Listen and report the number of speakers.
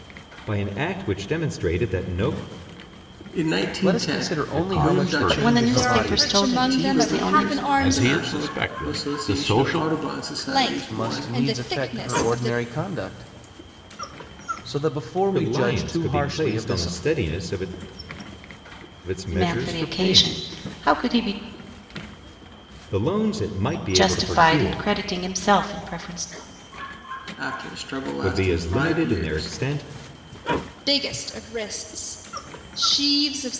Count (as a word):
six